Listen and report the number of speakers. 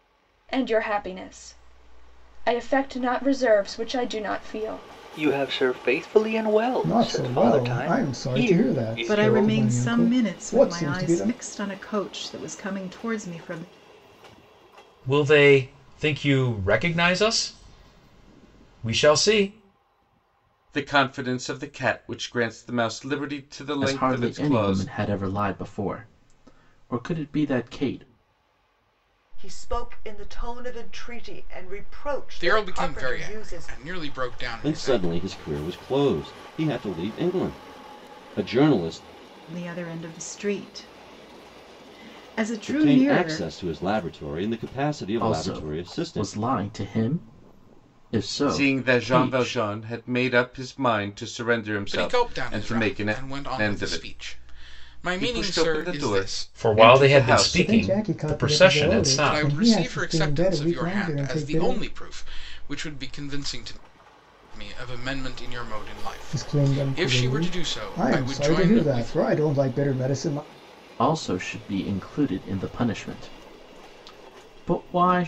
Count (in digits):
10